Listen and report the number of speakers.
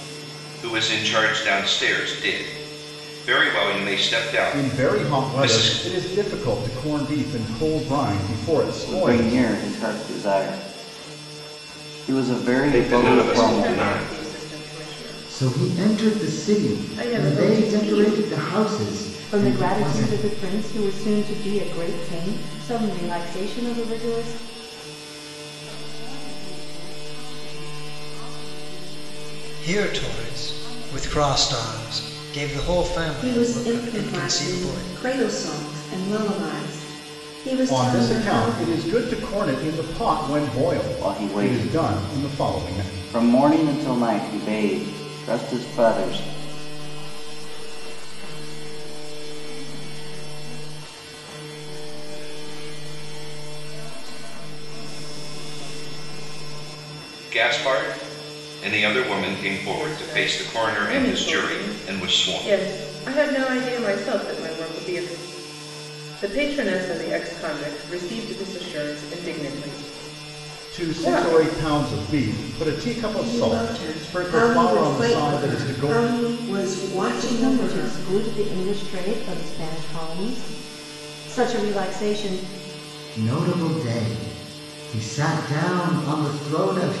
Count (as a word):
ten